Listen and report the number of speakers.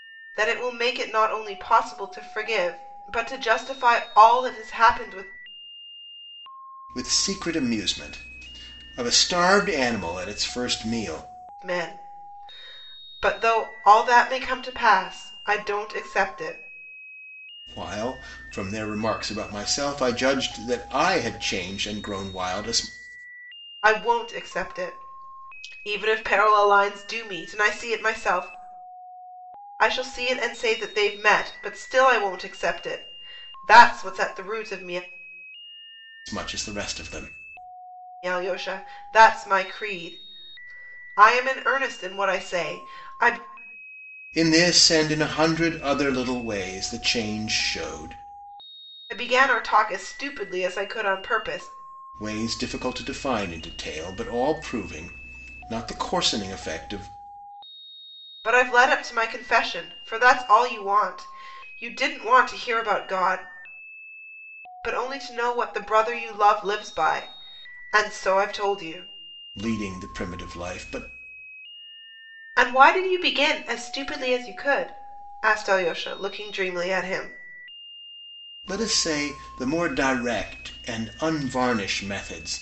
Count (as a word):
two